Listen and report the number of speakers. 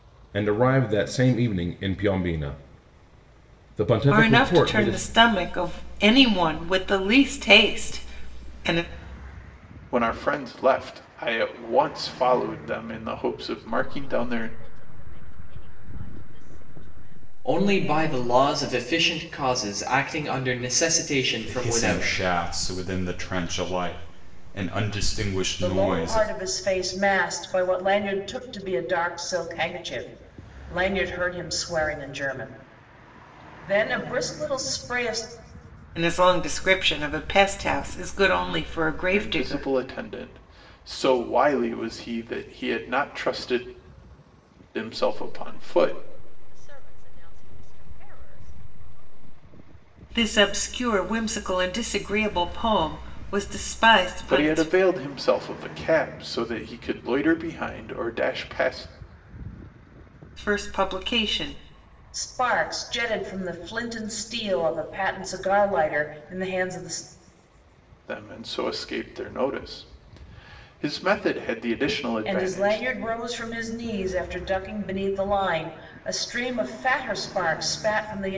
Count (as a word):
seven